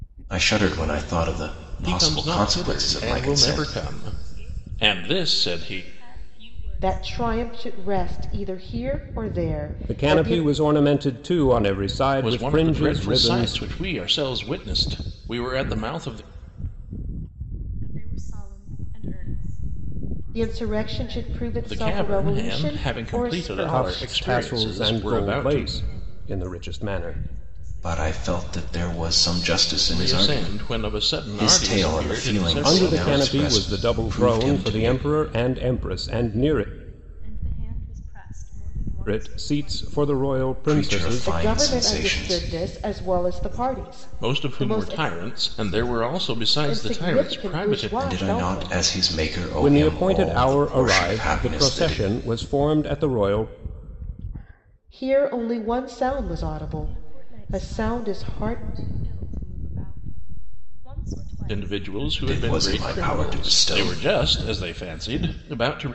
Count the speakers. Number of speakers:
five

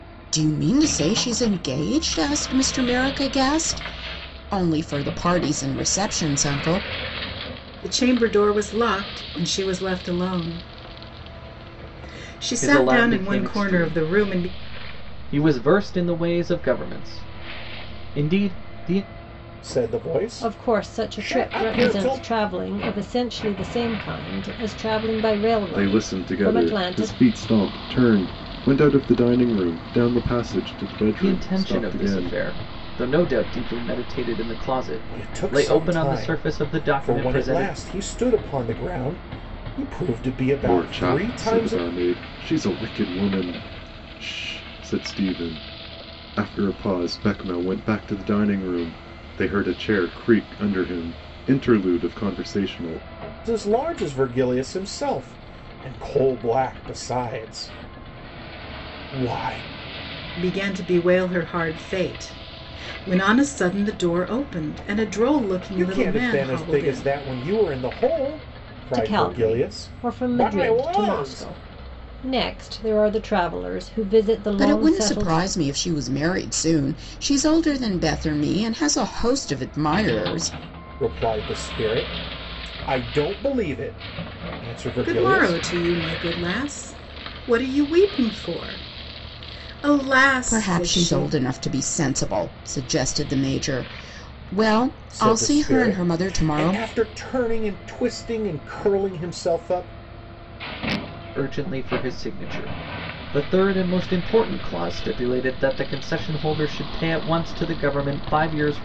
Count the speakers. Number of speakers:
six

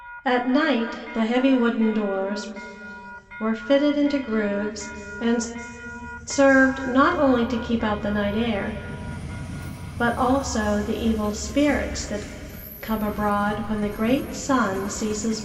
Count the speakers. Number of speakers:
one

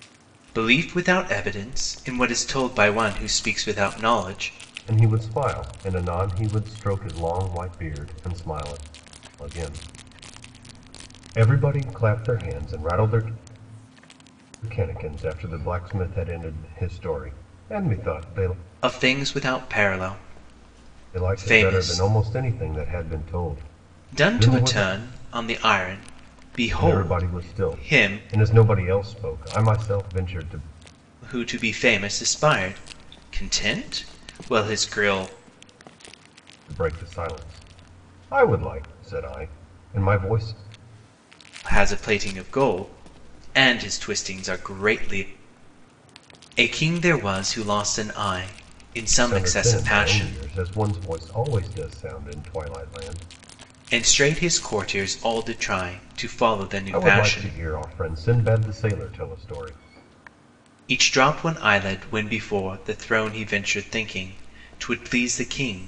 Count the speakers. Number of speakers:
two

